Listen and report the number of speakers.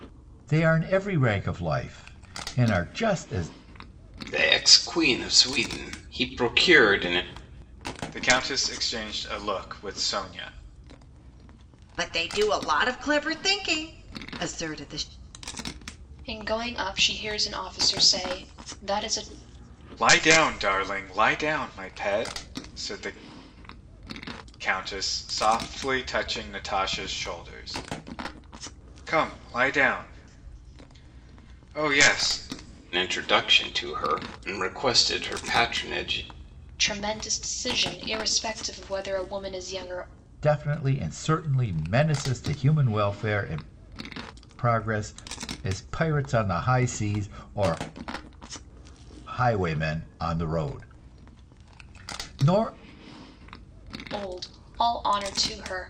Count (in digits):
5